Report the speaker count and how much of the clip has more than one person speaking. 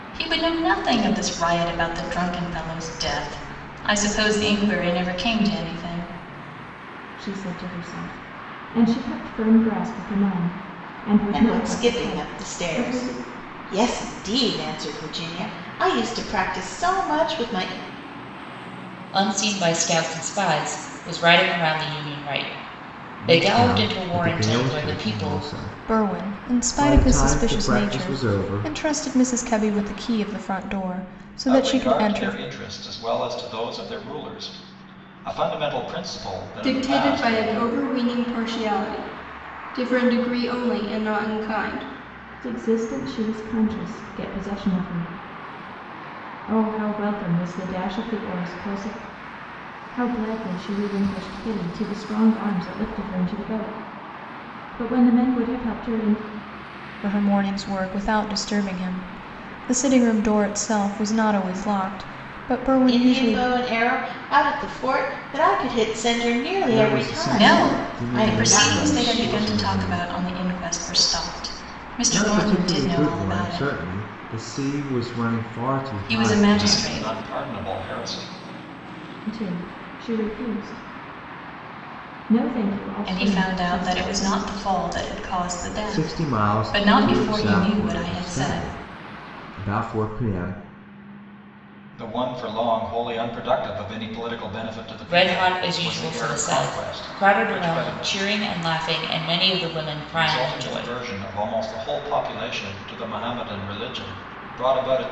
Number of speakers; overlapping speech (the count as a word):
eight, about 23%